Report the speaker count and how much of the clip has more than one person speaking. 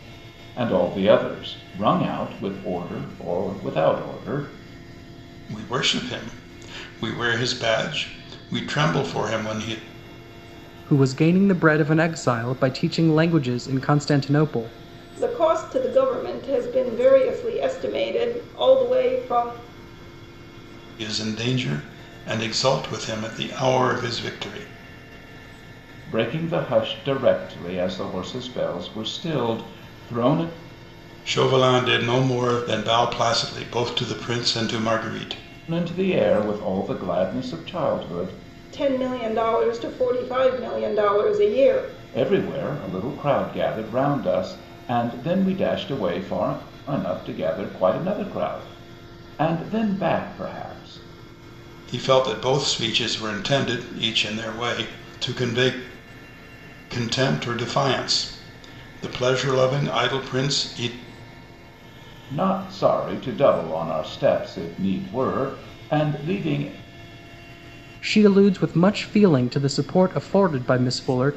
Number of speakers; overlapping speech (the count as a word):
four, no overlap